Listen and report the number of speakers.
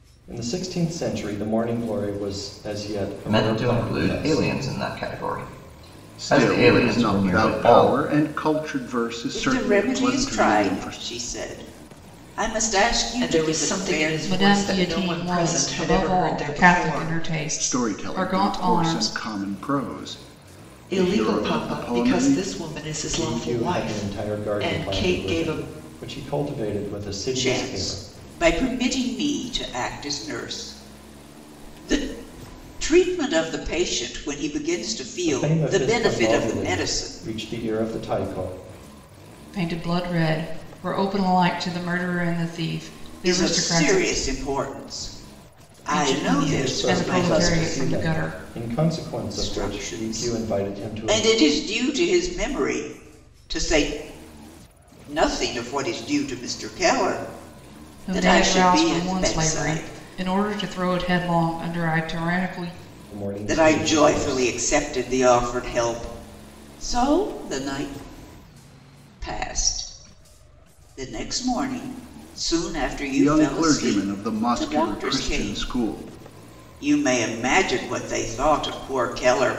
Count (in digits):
6